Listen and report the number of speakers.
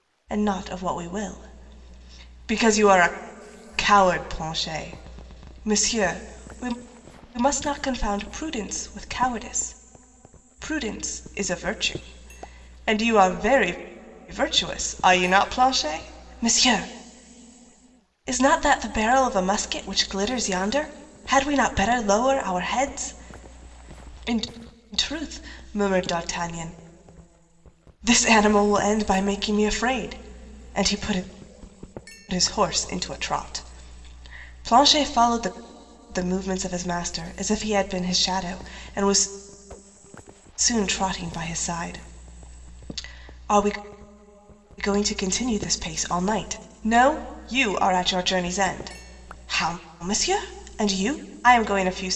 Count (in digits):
1